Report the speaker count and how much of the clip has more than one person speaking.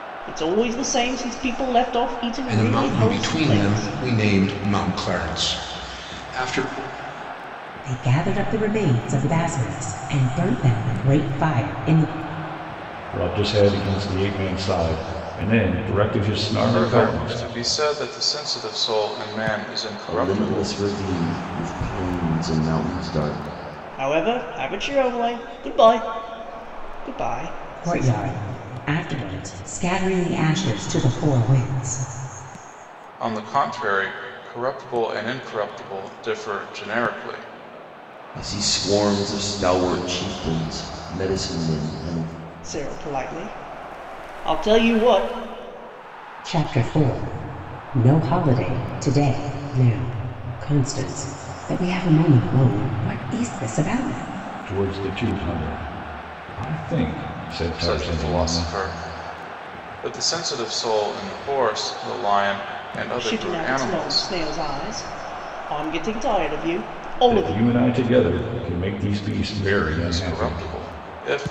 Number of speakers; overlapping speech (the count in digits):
6, about 9%